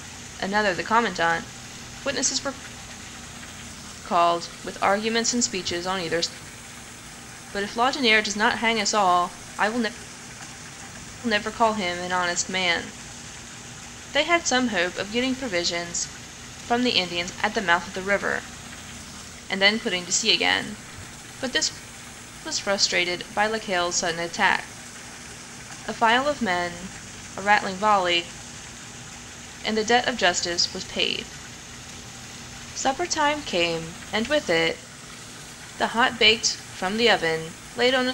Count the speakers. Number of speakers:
1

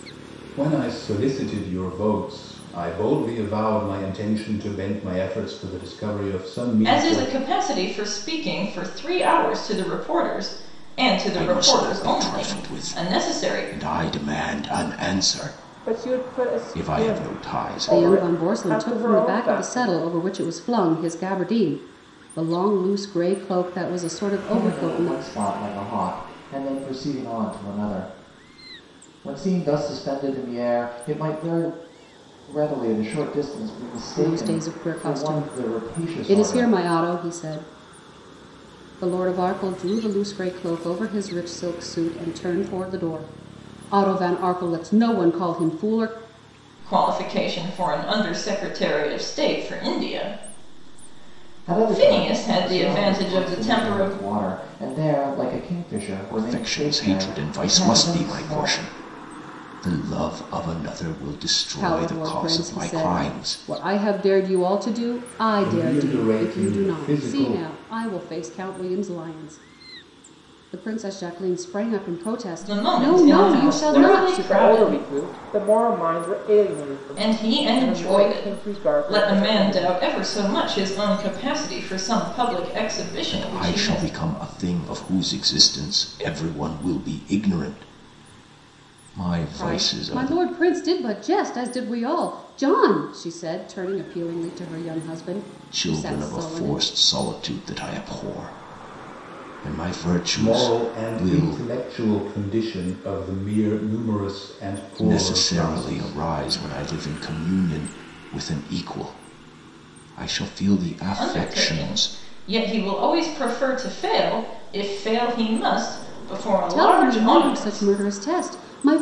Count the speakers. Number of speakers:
6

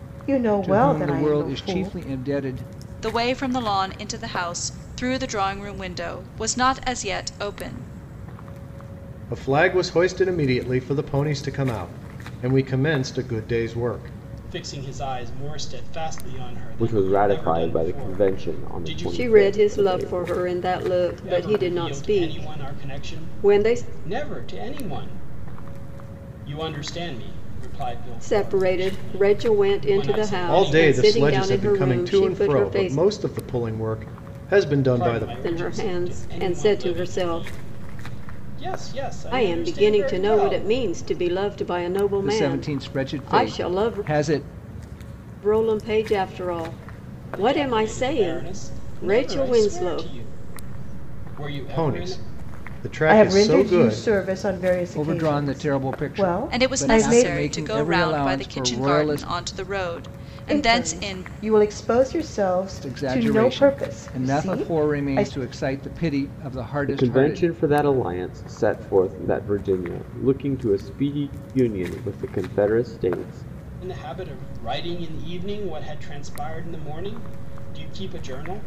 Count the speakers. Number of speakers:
7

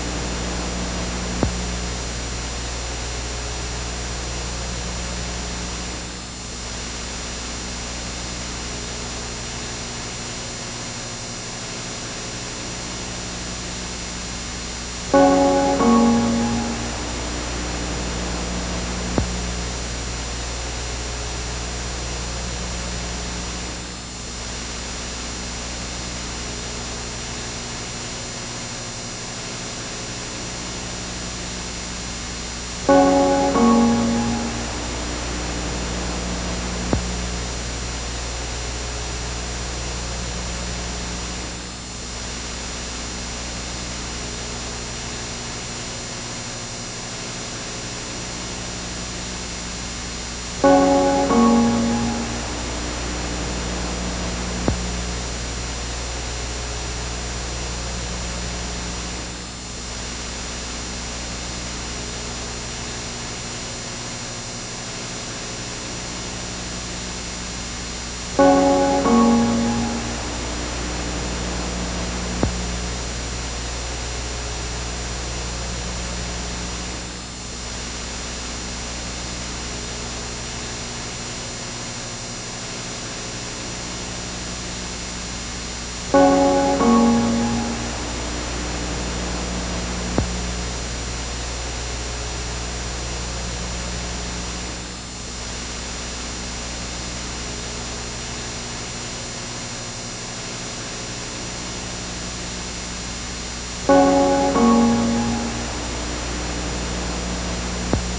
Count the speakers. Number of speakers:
0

